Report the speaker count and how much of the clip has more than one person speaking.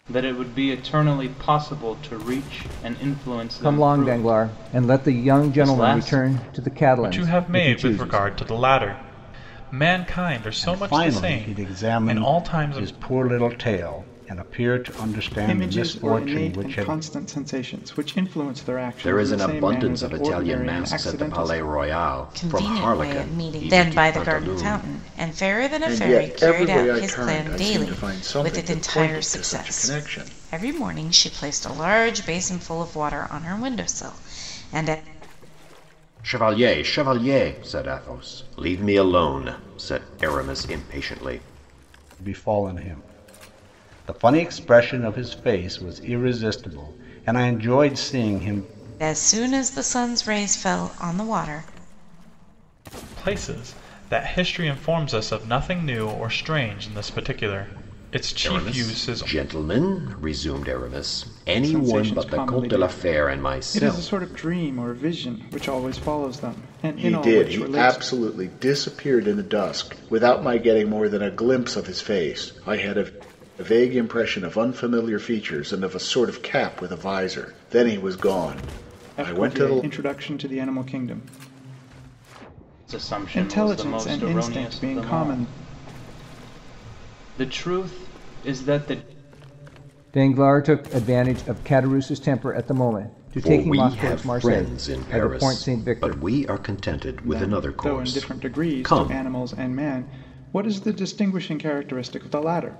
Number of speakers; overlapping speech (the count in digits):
8, about 30%